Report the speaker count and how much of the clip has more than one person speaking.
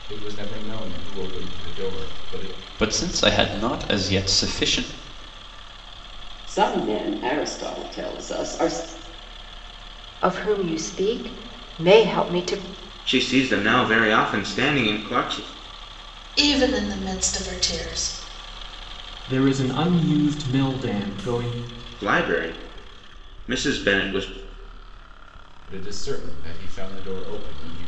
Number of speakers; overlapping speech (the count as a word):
seven, no overlap